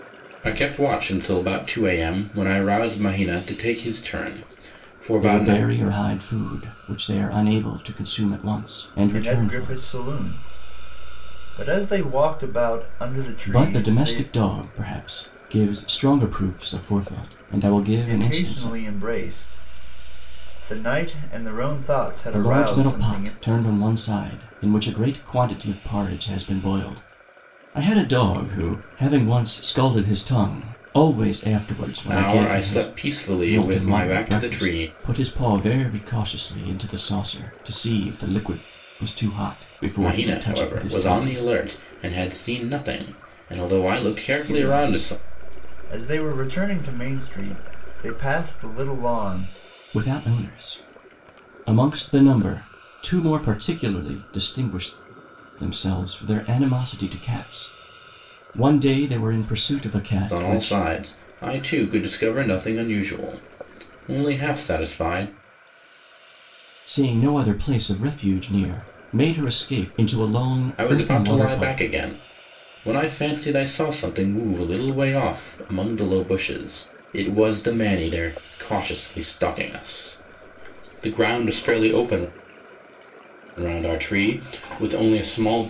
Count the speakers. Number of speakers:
3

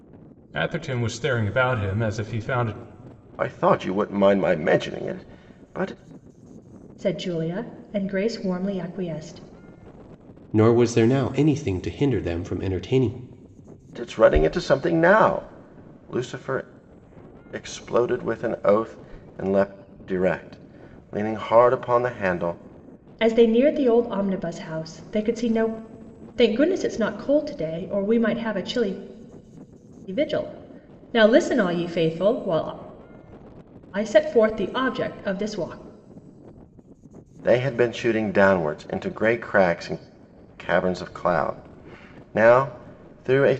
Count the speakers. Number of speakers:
4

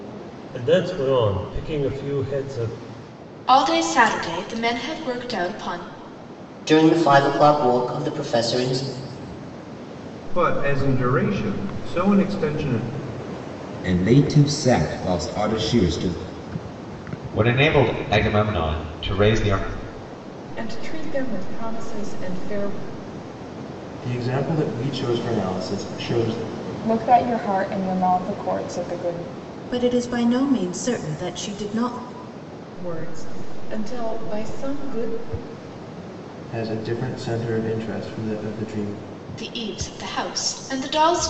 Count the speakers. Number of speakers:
10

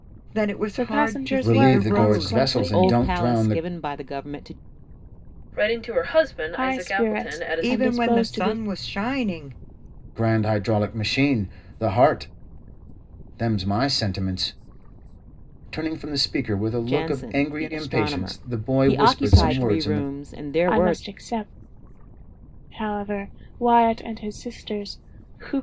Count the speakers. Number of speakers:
5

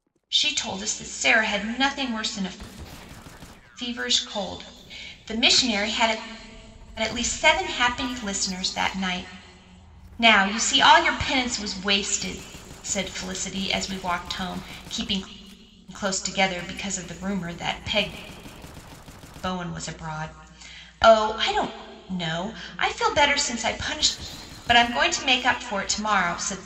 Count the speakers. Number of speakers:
1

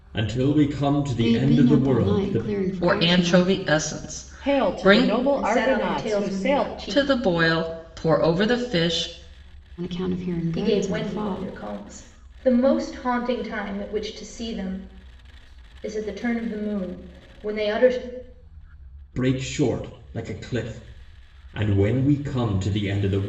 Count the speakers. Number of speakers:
5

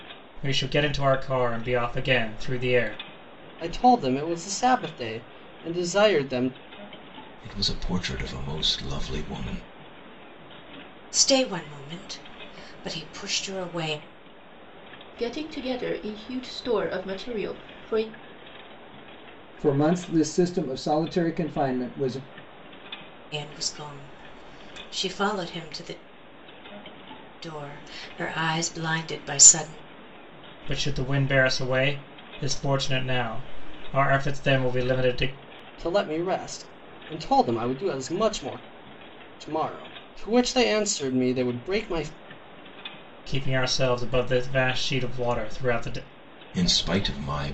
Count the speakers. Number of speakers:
6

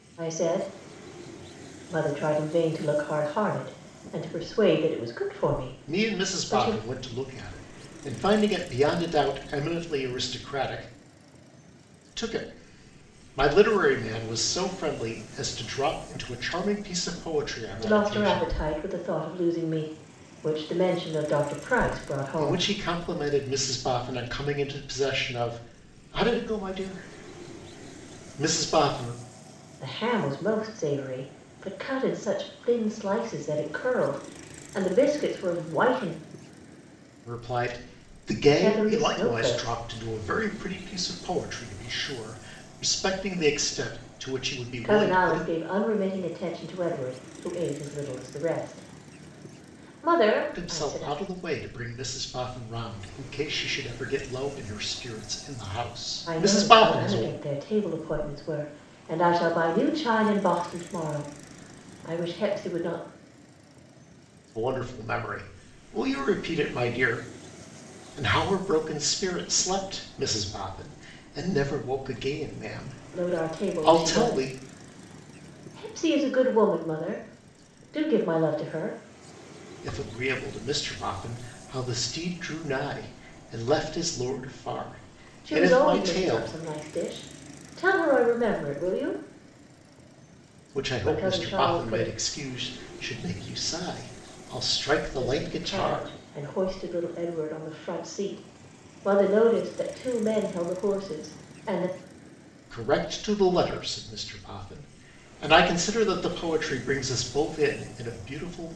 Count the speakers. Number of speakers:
2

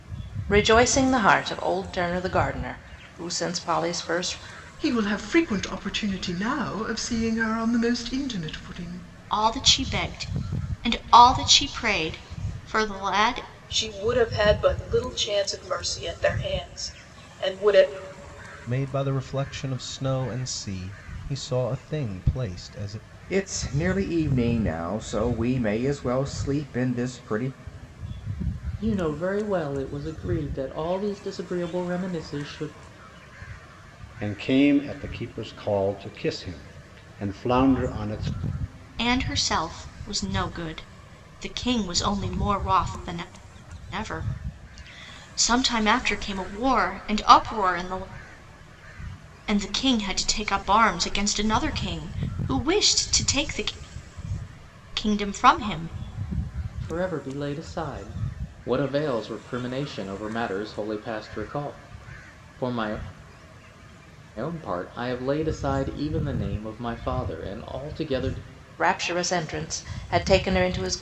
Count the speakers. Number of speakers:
8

